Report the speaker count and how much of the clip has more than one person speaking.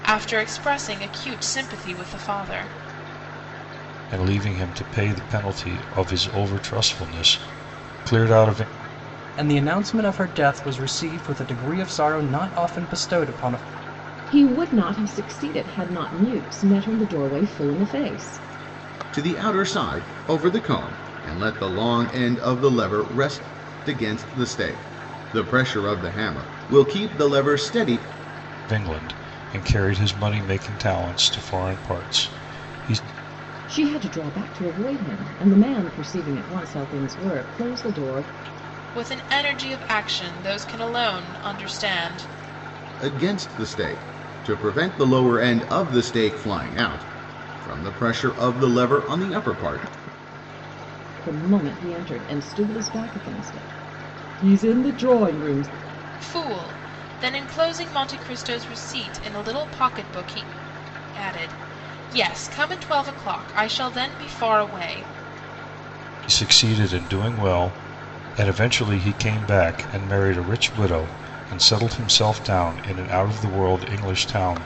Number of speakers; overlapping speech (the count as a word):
five, no overlap